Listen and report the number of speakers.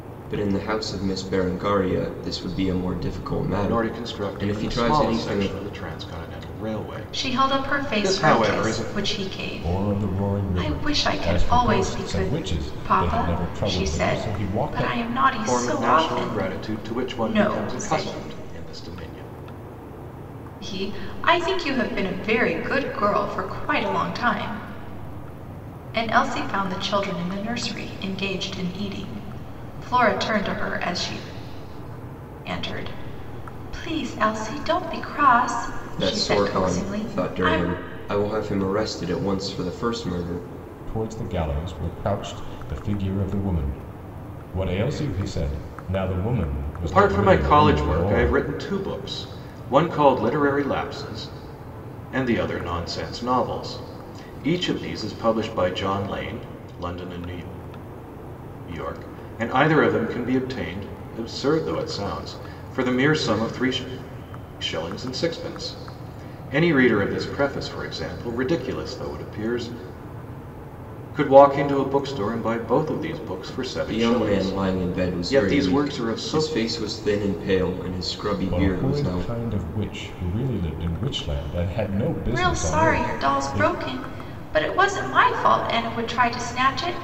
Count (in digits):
4